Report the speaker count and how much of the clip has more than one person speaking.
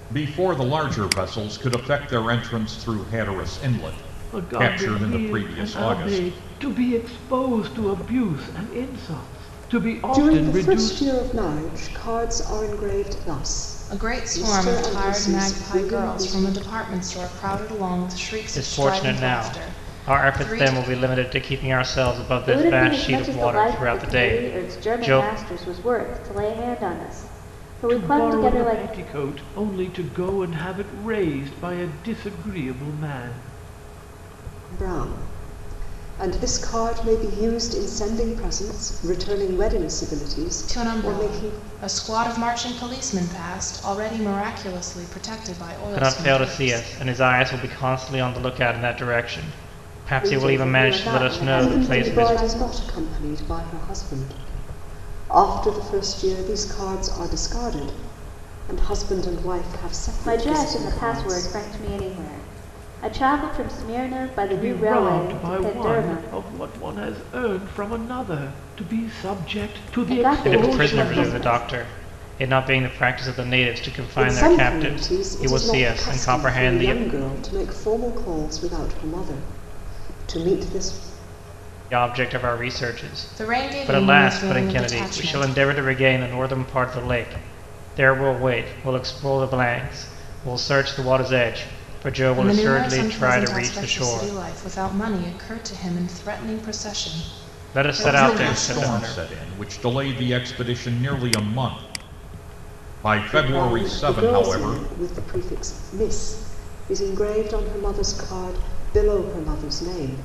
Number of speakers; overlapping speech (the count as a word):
six, about 29%